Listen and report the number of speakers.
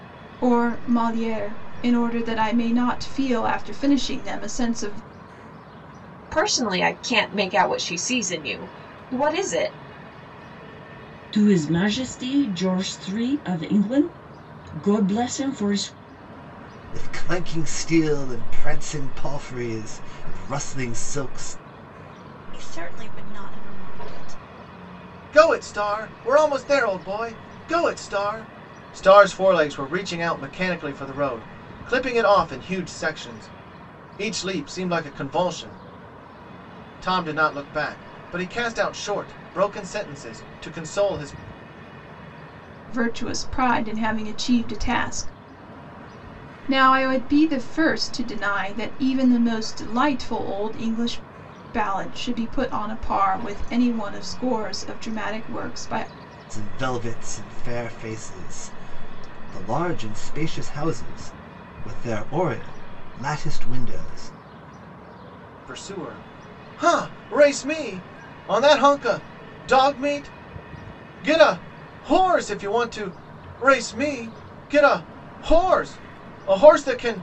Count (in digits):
6